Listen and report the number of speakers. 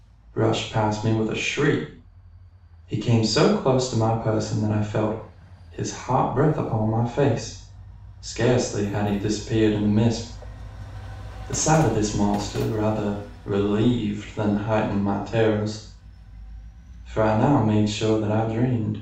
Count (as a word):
one